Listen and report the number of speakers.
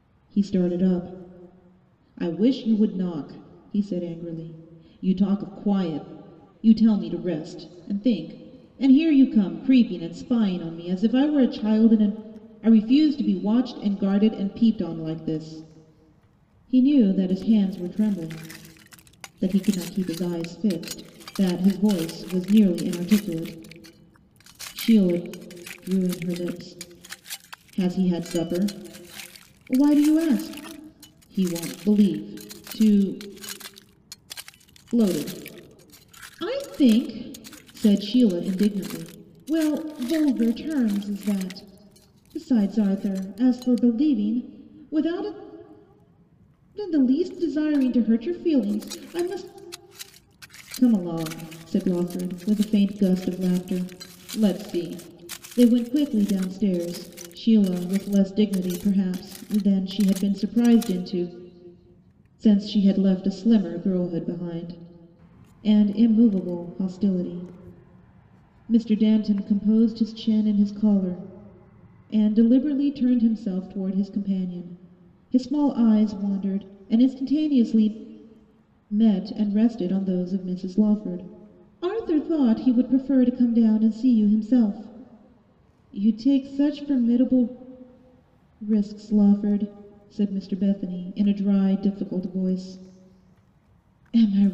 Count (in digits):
1